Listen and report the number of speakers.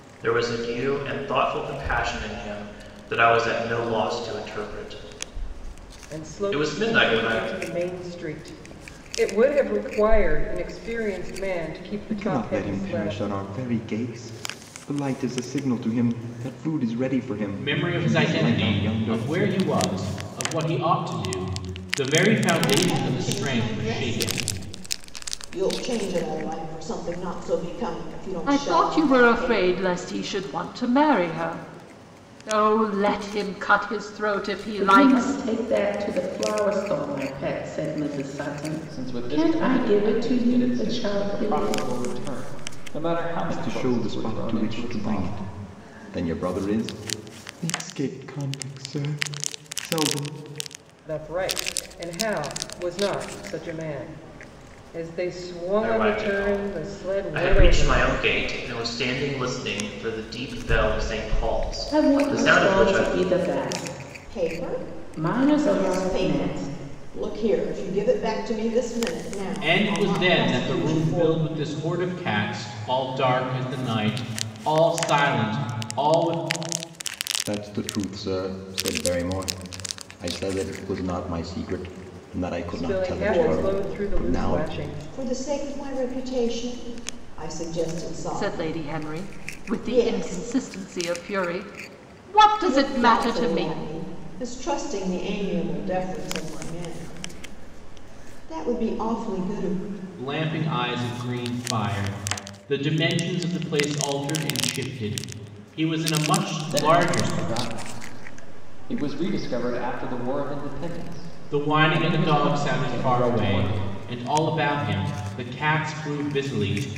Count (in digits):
8